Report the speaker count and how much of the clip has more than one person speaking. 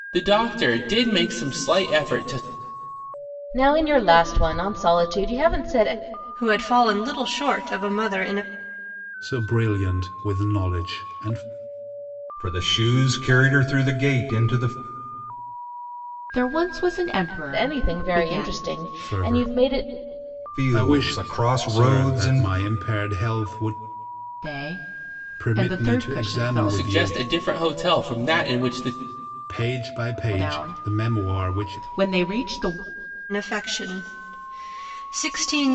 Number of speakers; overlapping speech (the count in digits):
6, about 19%